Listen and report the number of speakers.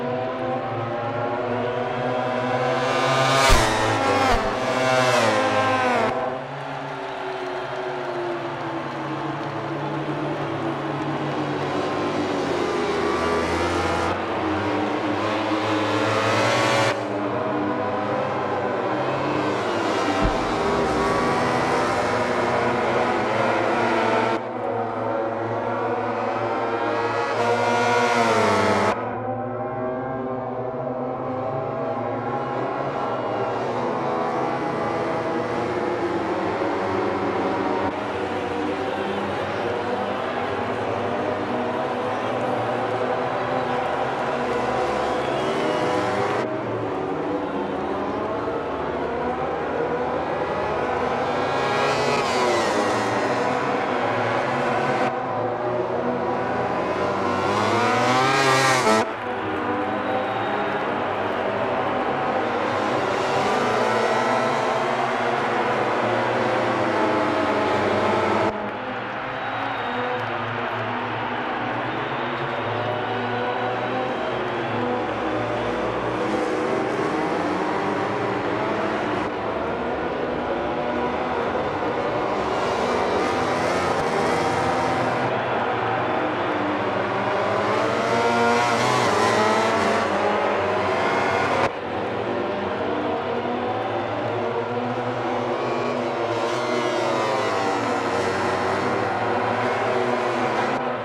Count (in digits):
0